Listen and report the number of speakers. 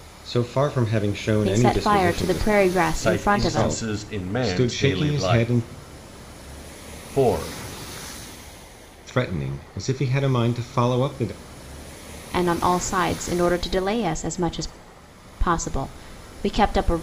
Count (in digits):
3